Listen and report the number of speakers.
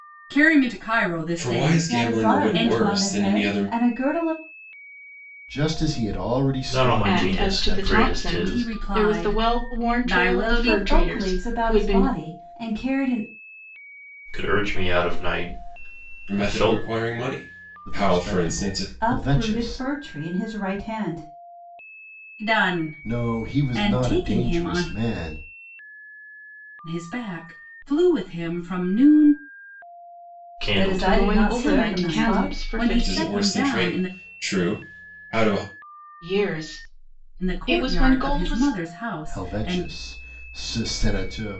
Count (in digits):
6